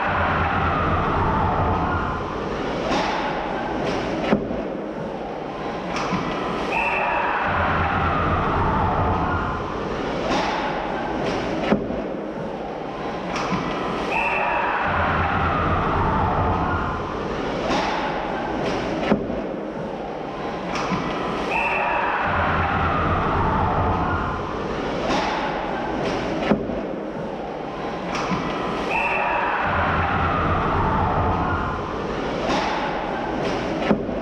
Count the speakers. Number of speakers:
zero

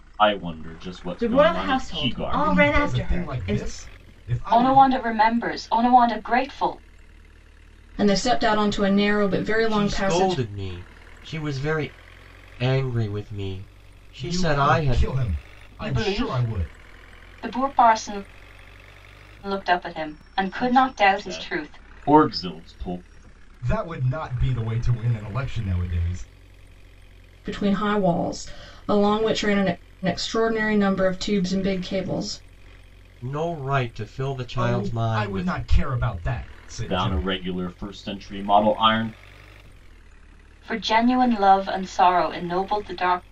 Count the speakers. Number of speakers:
six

